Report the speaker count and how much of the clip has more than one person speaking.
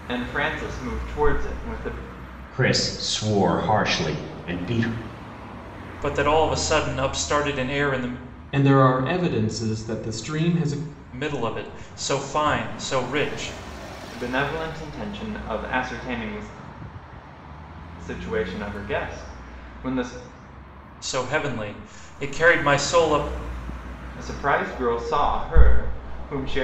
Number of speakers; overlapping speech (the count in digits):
4, no overlap